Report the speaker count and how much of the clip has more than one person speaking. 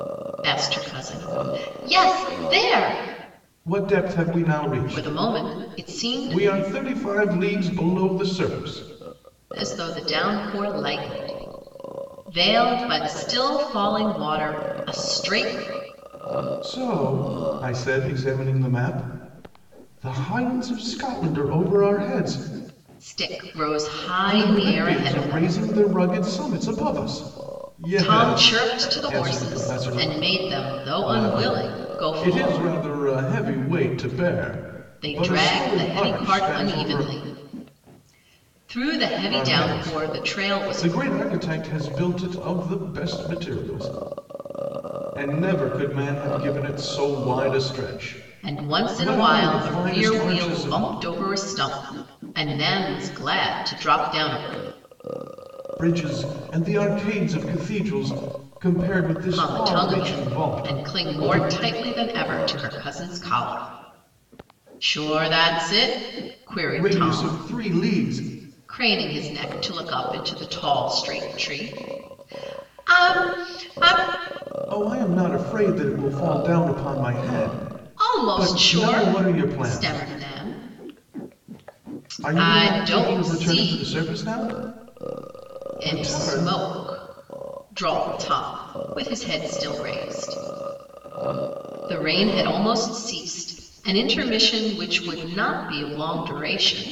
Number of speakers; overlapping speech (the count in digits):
2, about 22%